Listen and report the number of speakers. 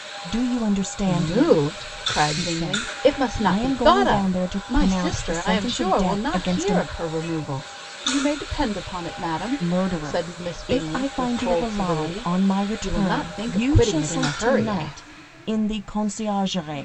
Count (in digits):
2